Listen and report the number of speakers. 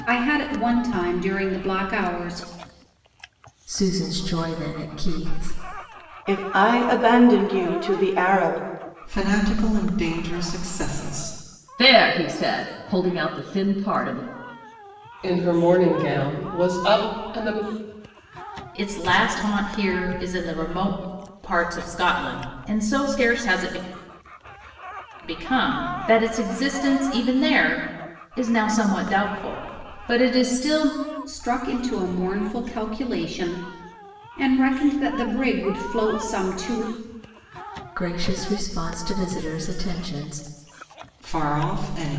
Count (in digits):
7